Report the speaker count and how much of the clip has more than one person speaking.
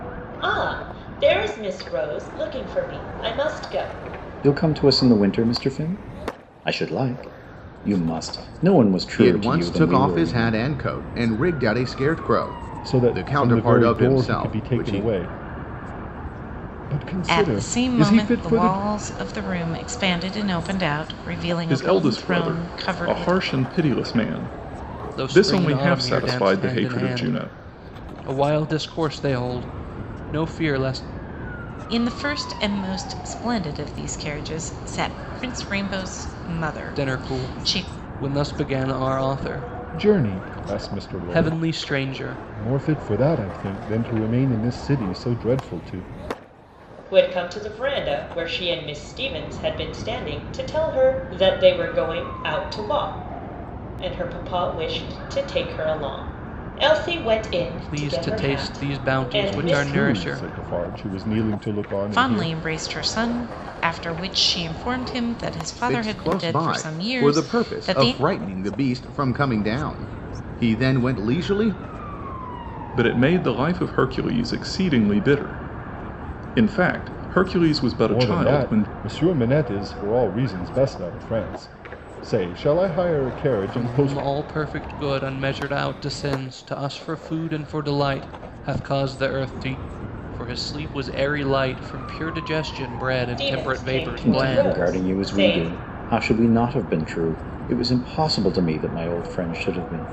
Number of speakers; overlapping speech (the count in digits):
7, about 23%